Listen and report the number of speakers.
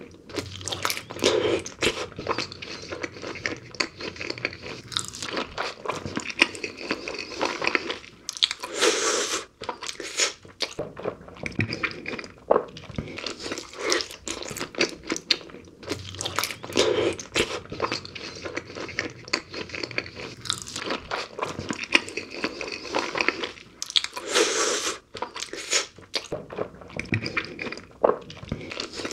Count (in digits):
0